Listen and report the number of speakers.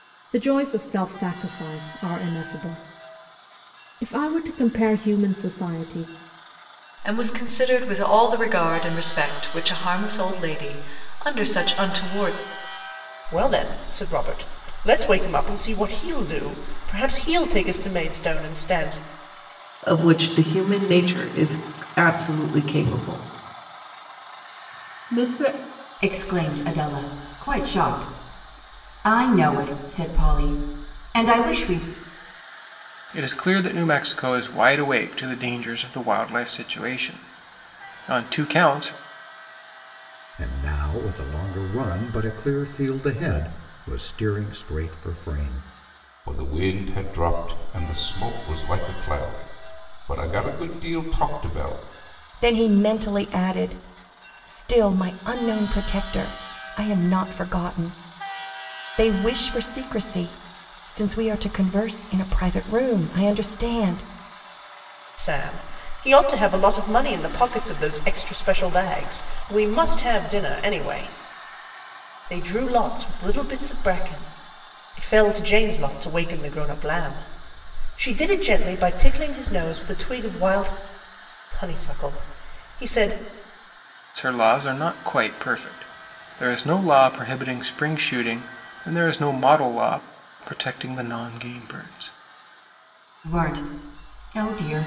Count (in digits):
9